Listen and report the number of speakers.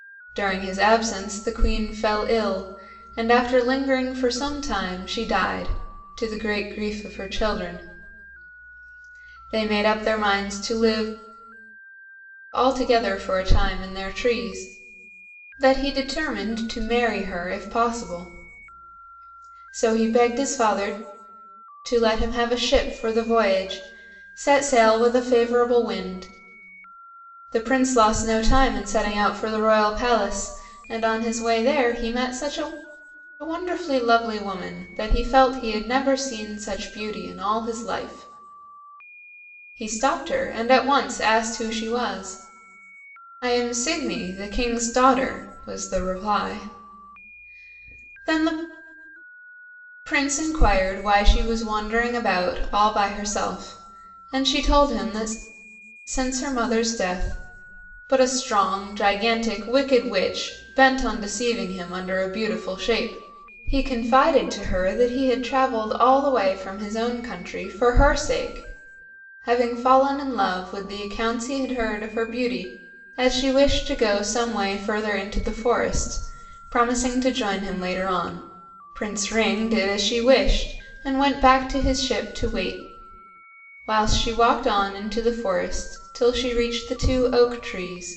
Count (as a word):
one